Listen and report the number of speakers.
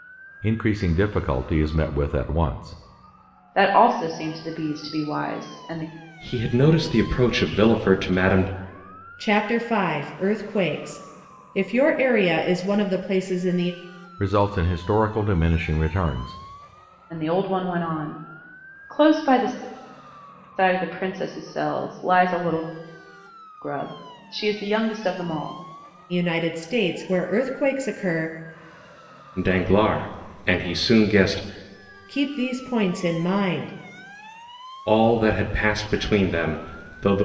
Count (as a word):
four